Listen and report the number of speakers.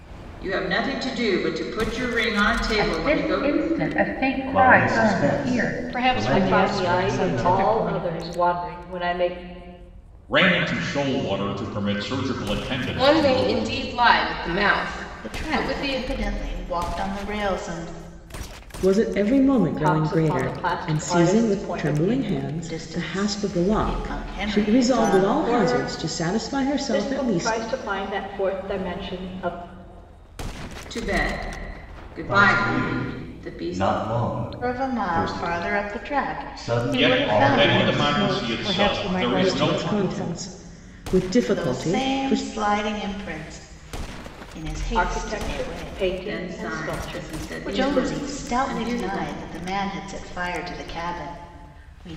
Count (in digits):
9